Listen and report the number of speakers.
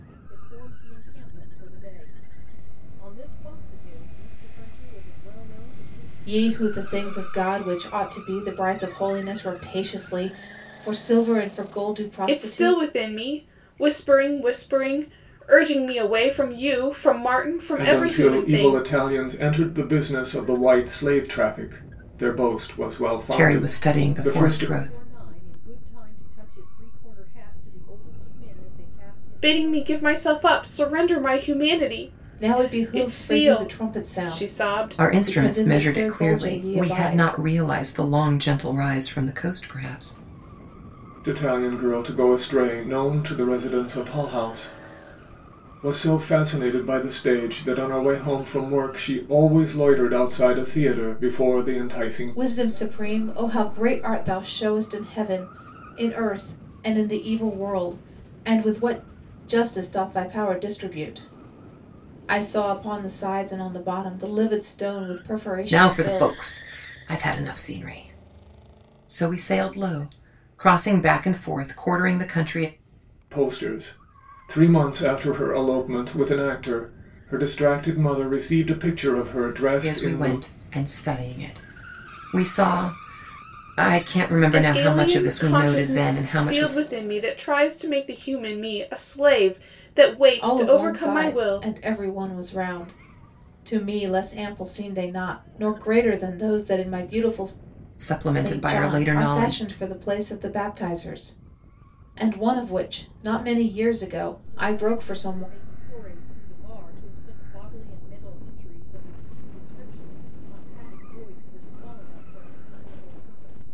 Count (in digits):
5